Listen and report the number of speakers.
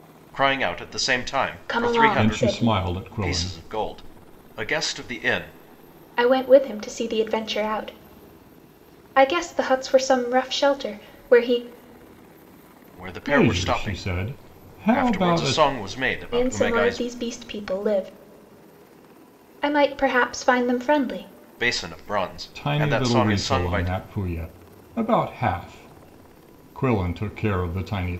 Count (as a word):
three